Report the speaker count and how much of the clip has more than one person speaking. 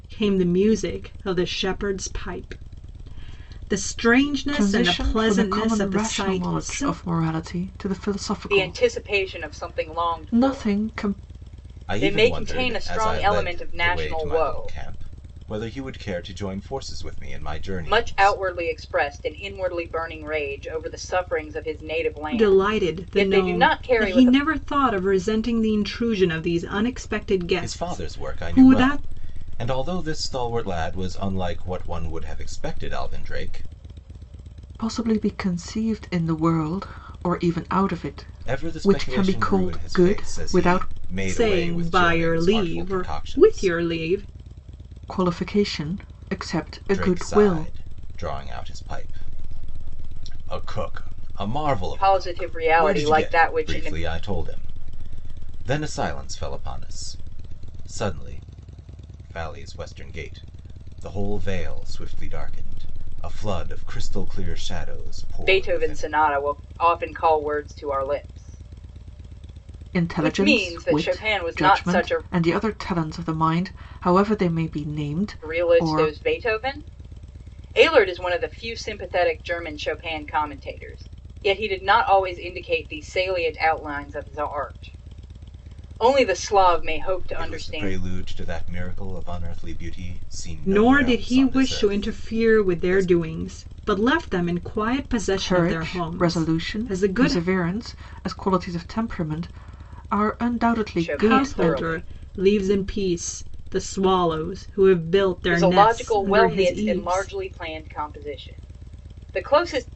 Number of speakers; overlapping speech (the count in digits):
4, about 30%